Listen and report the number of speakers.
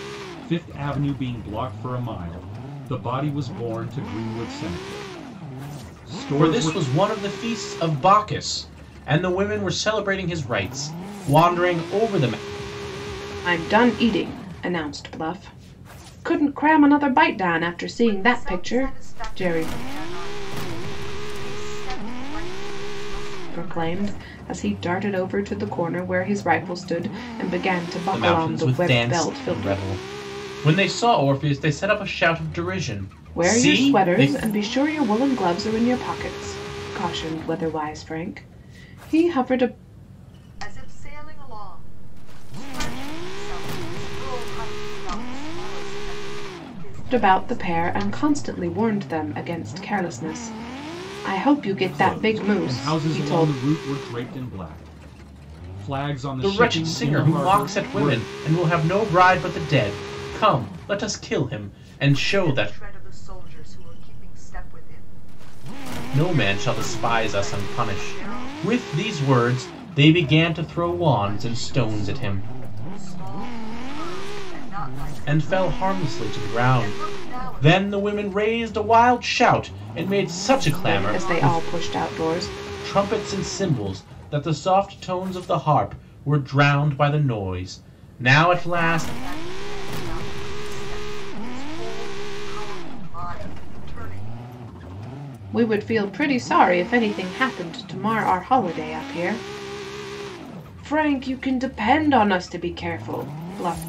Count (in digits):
4